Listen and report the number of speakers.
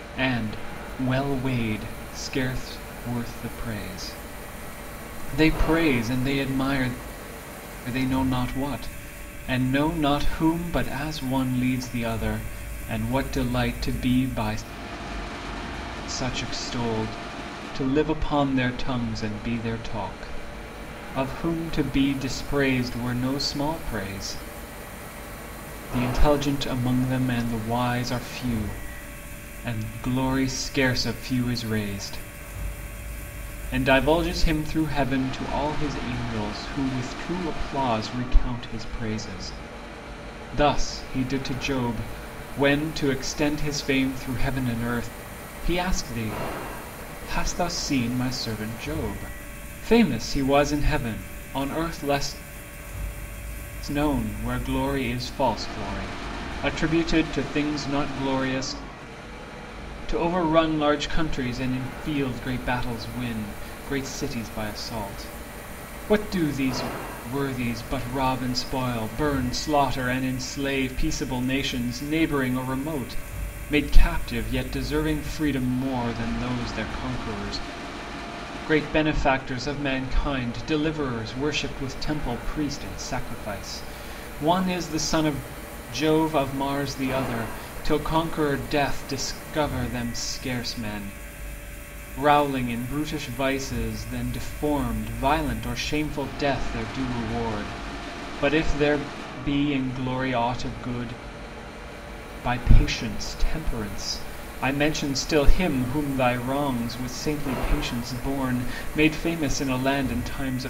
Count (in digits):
1